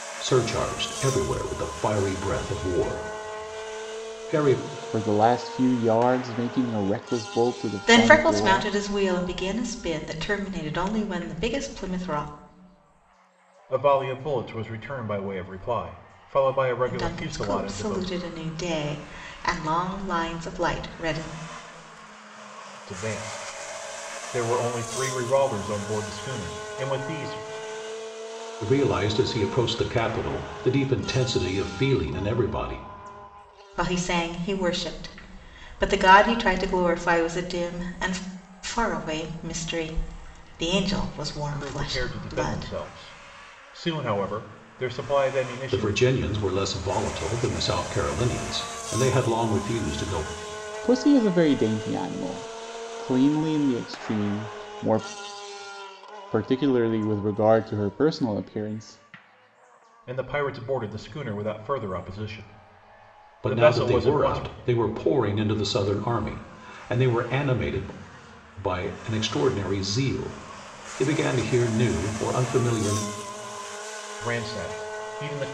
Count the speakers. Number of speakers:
4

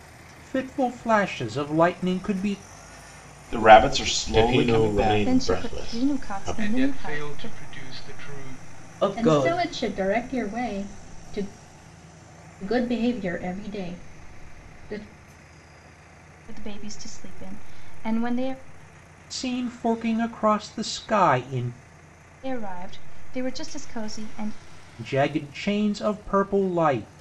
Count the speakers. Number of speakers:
7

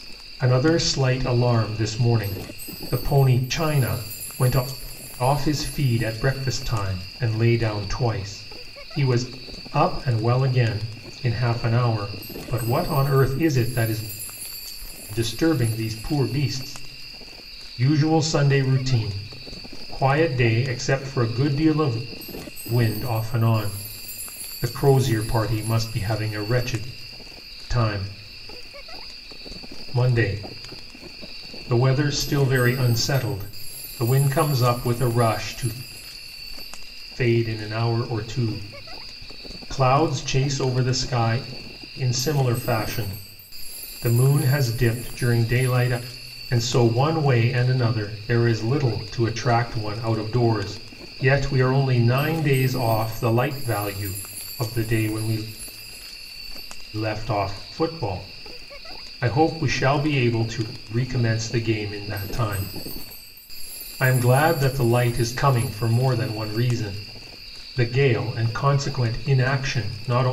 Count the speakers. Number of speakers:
1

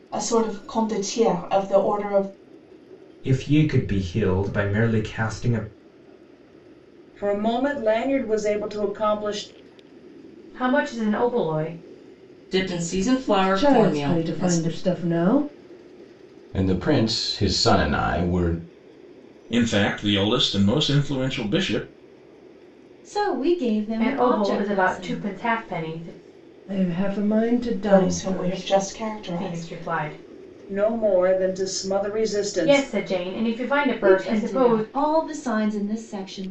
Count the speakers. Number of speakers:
9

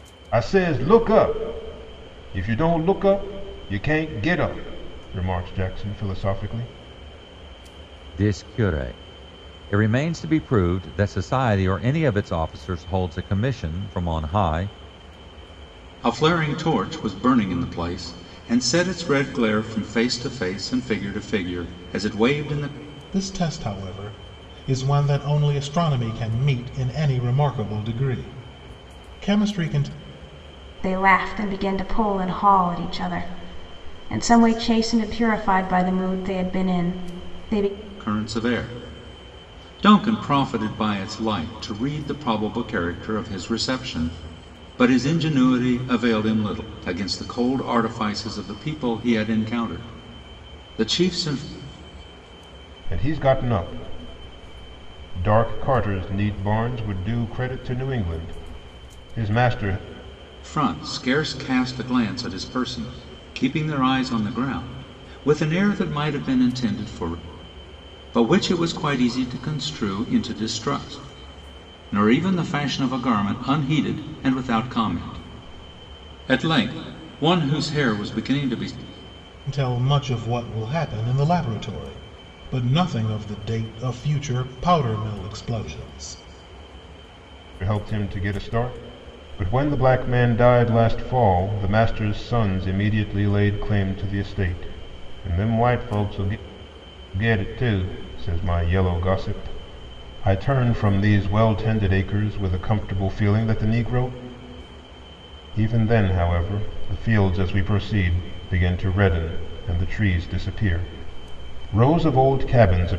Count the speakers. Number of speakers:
5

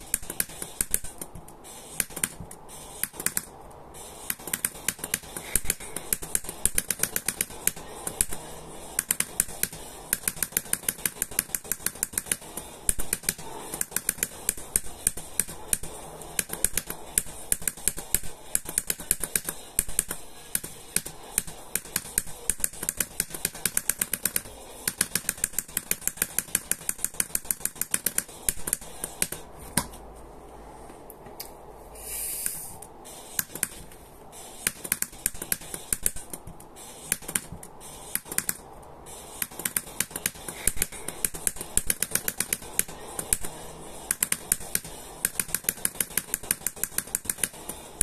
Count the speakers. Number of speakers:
0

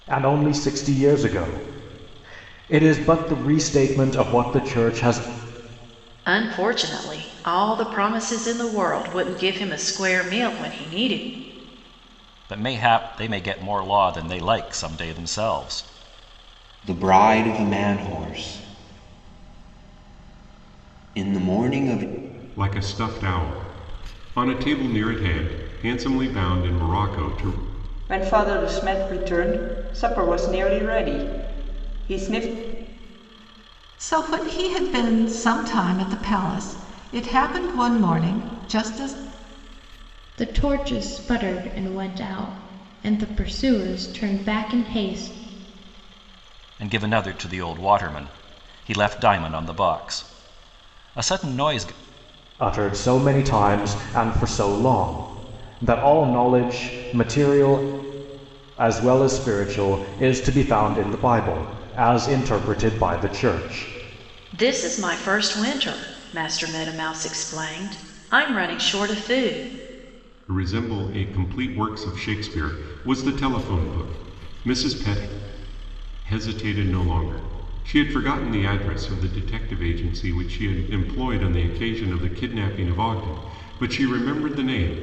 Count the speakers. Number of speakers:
8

